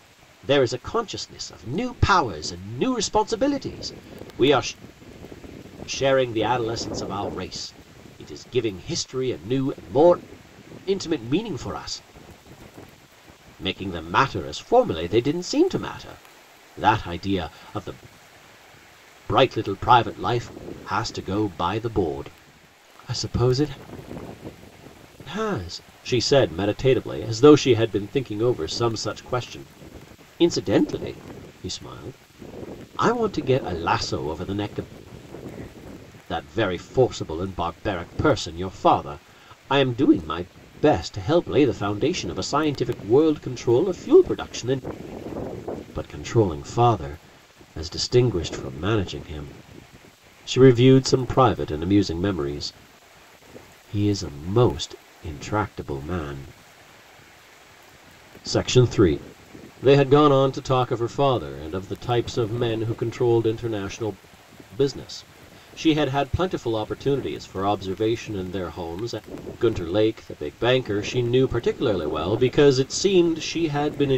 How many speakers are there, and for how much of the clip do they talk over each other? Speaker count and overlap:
one, no overlap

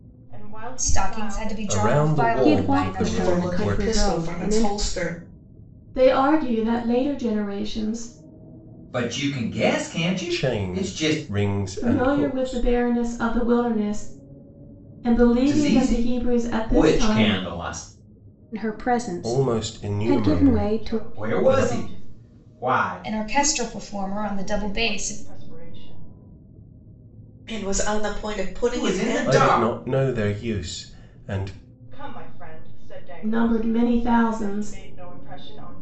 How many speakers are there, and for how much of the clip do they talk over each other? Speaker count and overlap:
seven, about 42%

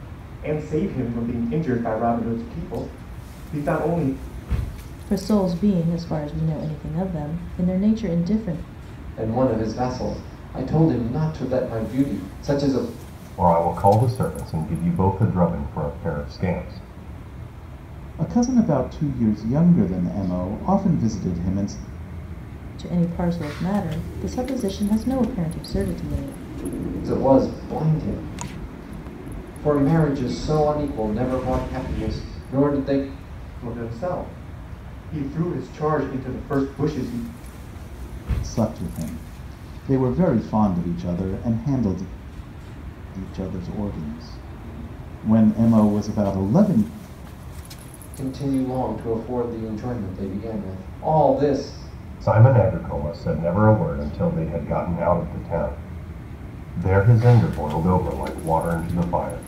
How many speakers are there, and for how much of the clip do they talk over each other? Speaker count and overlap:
five, no overlap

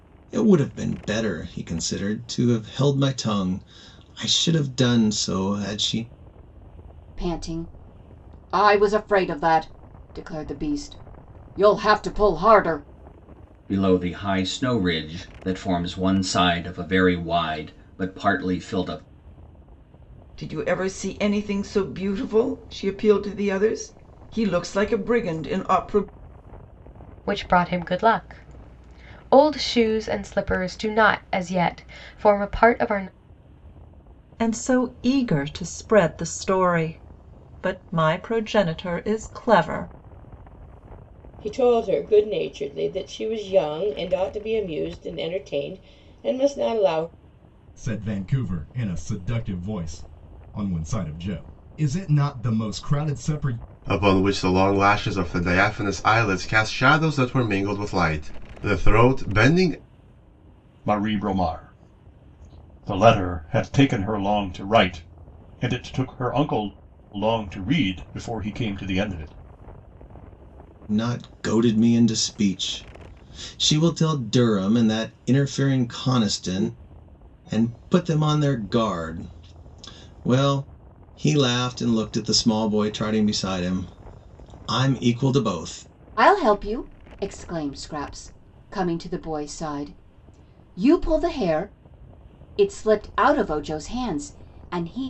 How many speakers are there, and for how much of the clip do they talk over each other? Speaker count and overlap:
ten, no overlap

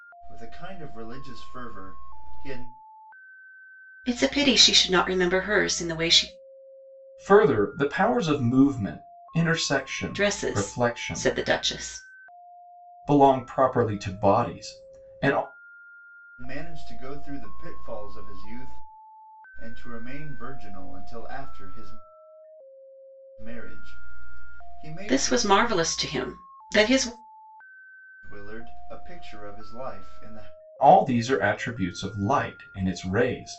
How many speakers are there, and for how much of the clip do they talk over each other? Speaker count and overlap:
three, about 6%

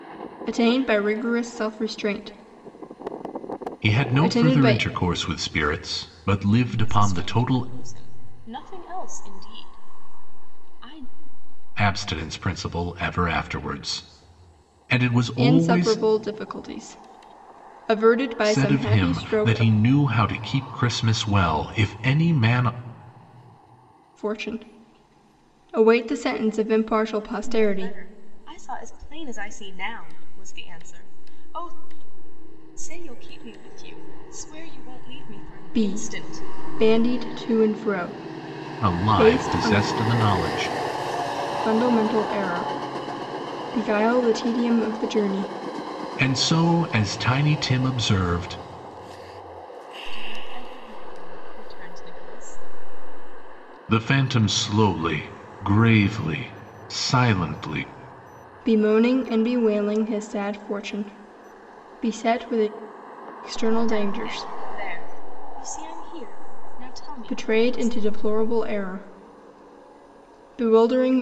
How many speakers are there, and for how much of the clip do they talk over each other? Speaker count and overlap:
three, about 11%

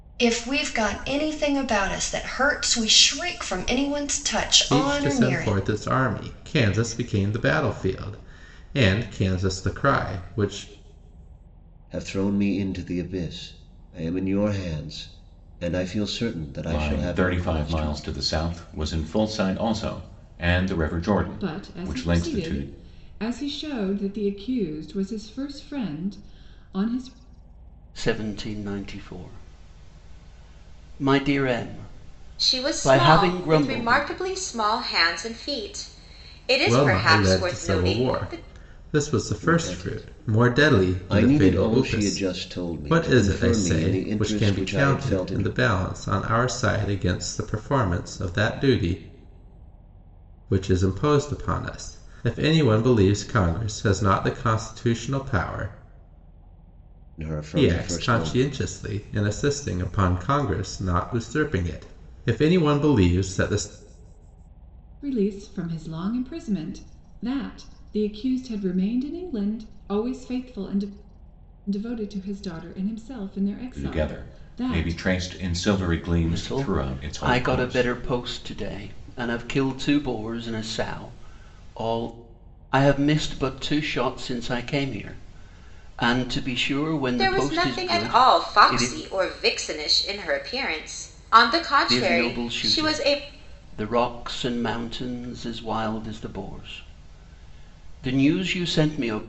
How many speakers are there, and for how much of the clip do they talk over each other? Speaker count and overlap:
seven, about 20%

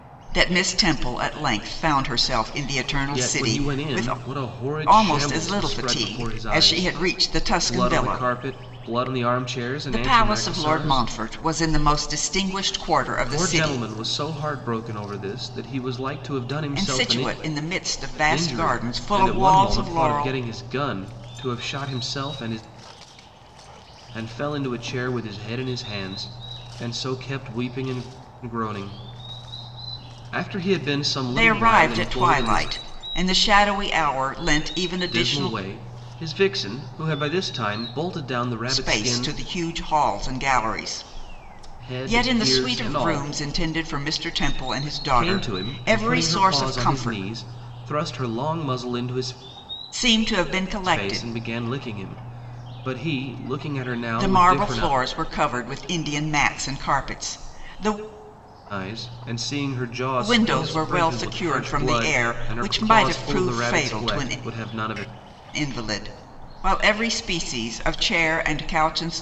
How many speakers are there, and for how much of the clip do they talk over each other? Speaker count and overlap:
two, about 29%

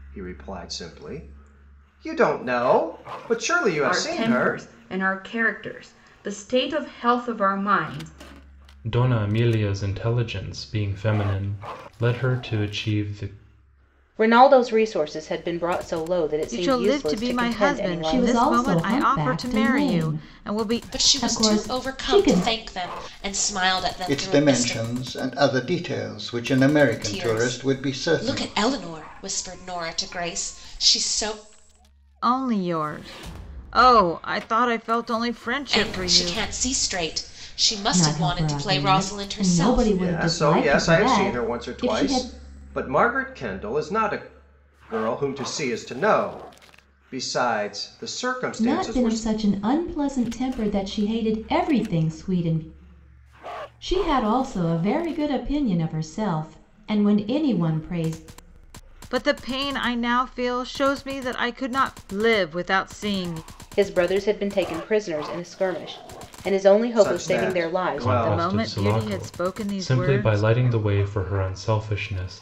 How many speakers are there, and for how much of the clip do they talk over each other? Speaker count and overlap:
eight, about 25%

